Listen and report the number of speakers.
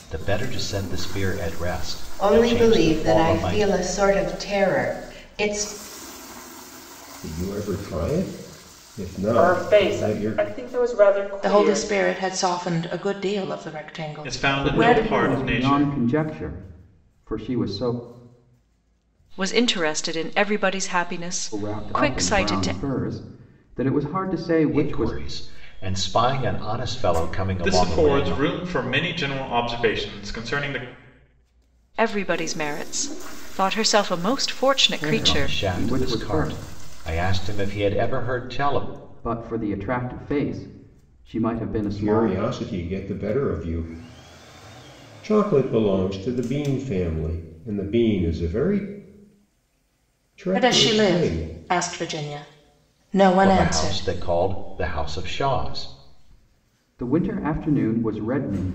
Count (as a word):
eight